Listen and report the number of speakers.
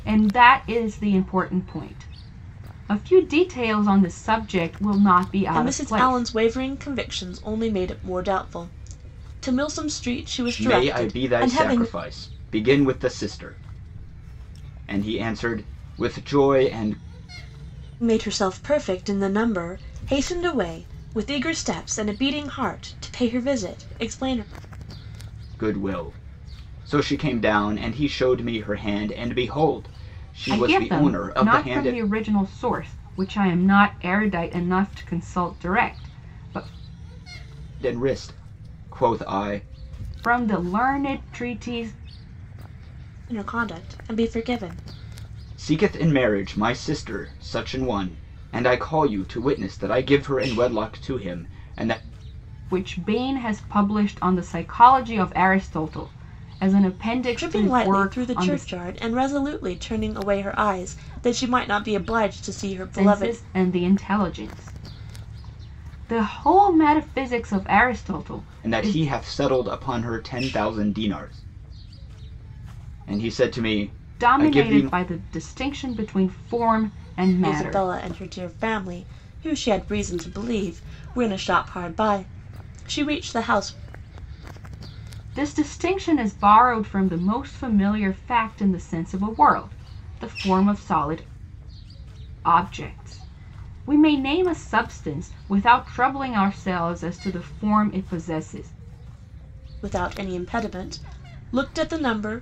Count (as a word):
three